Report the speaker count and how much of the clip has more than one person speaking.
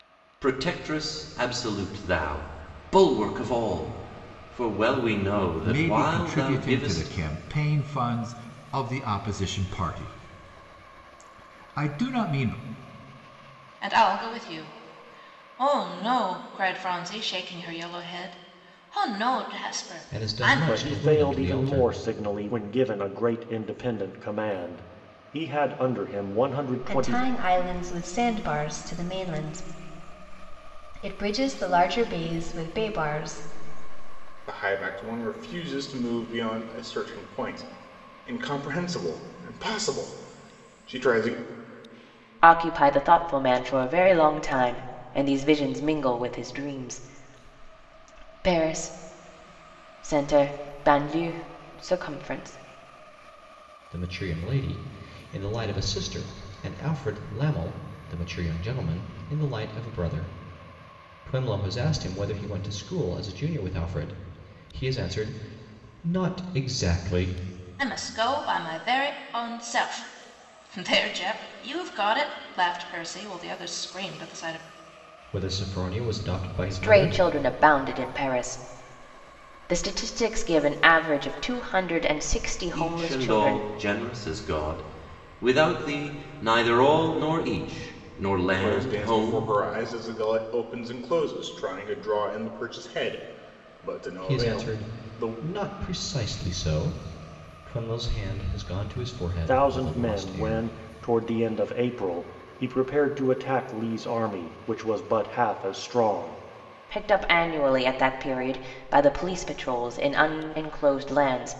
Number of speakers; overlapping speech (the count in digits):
8, about 8%